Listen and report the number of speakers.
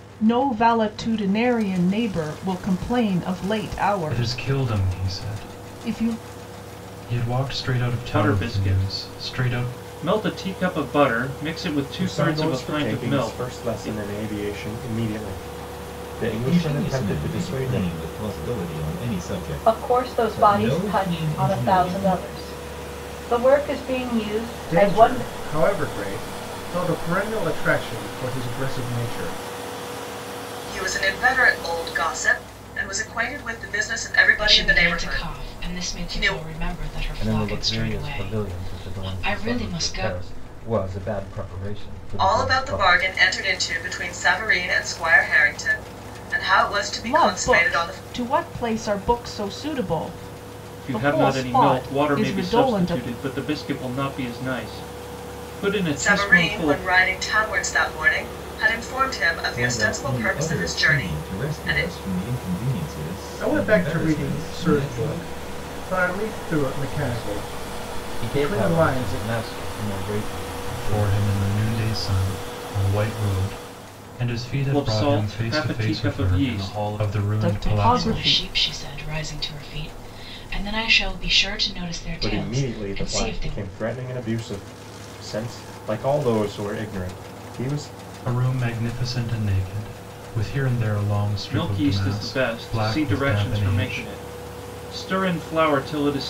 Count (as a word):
ten